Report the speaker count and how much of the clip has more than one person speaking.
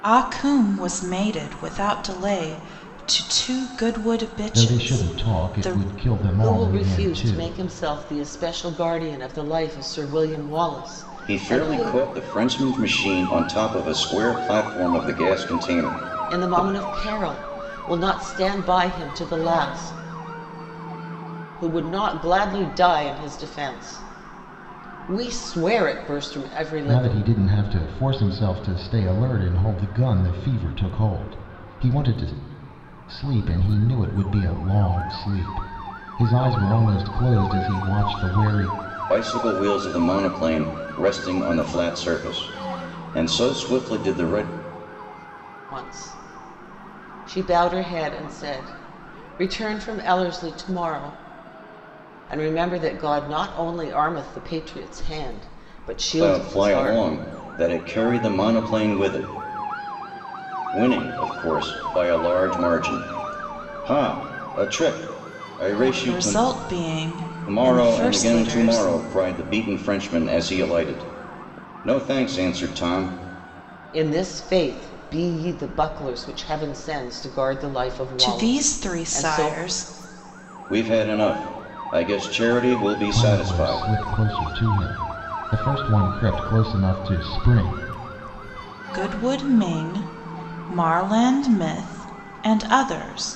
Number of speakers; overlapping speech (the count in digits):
4, about 10%